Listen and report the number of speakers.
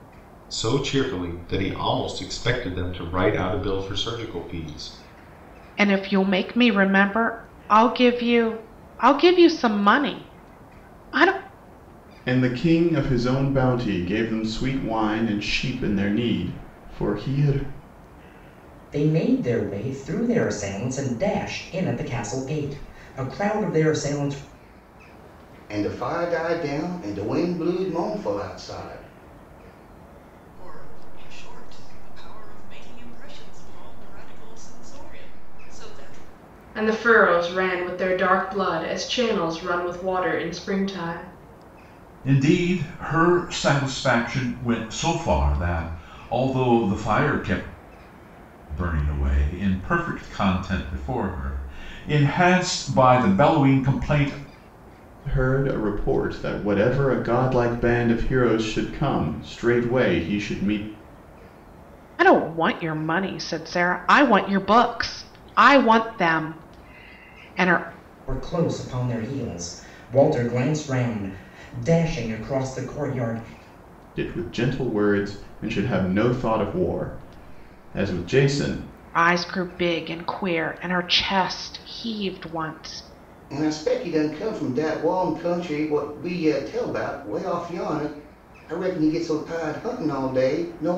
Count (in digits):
8